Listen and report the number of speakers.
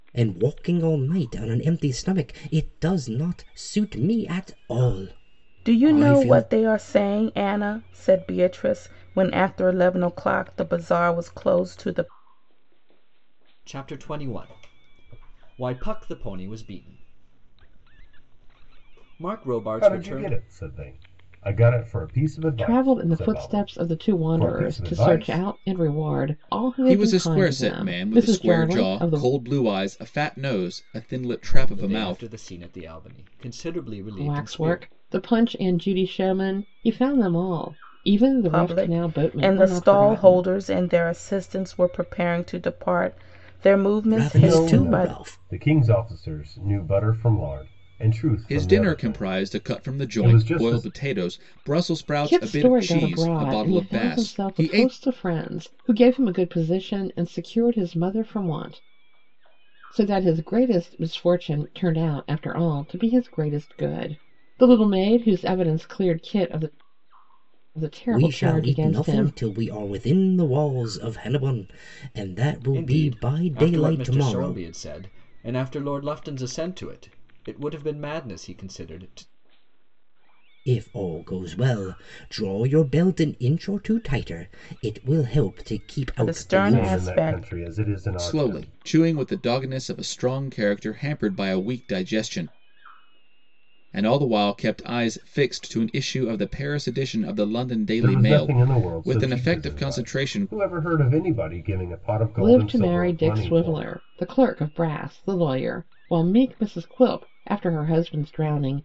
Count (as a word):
six